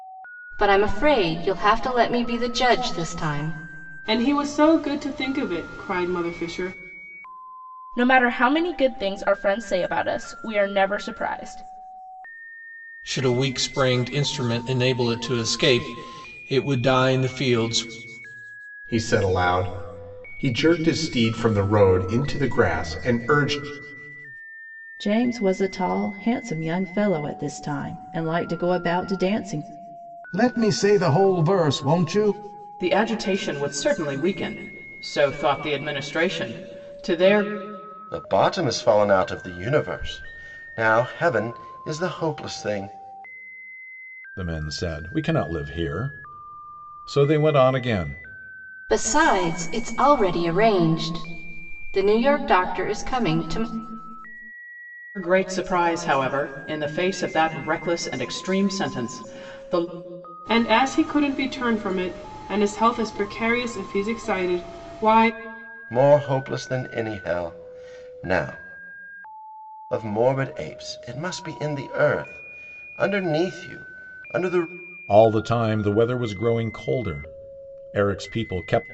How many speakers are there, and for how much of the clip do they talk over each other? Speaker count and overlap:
10, no overlap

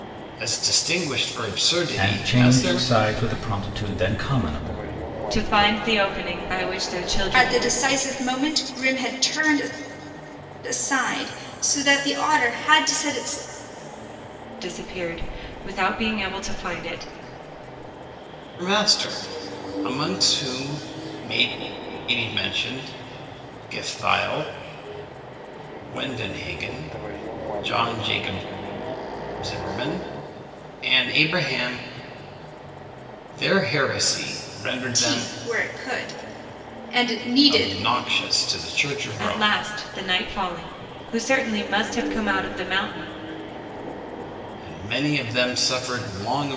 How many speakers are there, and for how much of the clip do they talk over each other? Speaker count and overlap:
4, about 5%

